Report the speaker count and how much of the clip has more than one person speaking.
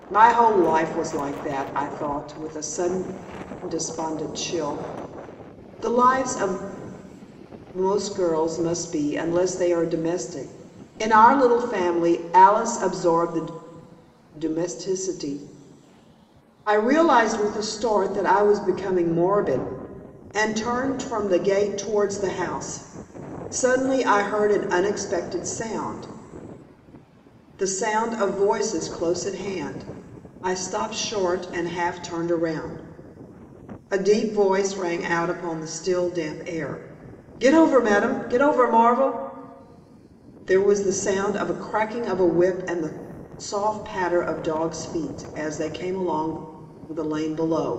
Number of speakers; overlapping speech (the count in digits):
1, no overlap